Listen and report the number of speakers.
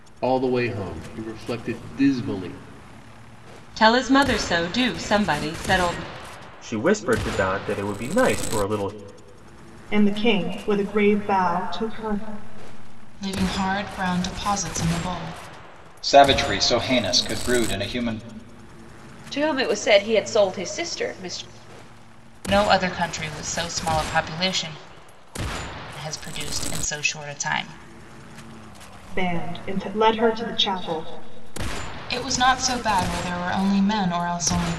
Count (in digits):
8